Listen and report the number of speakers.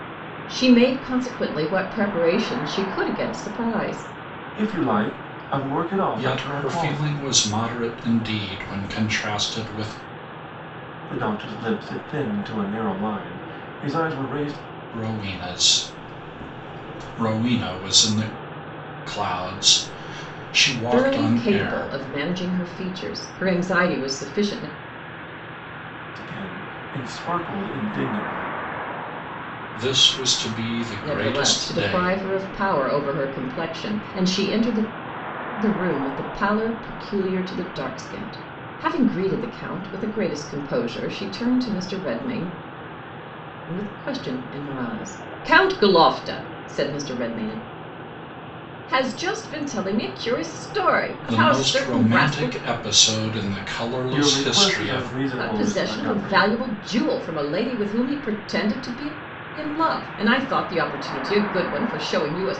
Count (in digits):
3